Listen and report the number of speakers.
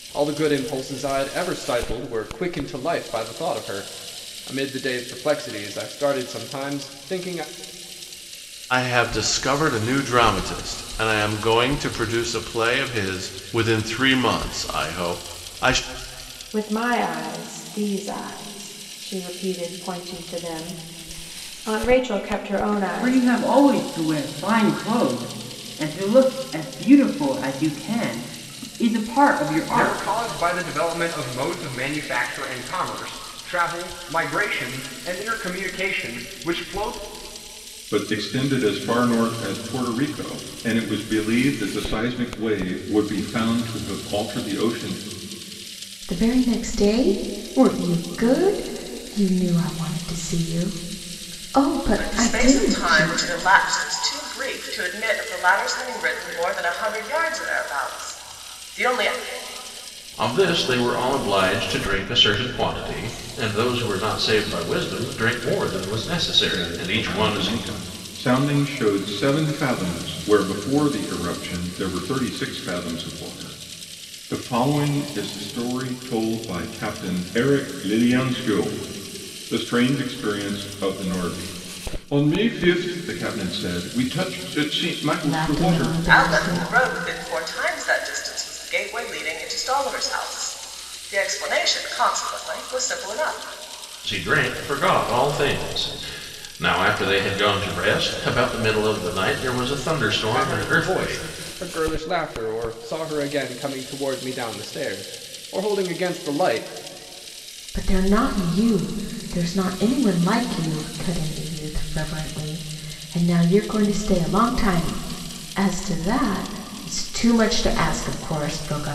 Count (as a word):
nine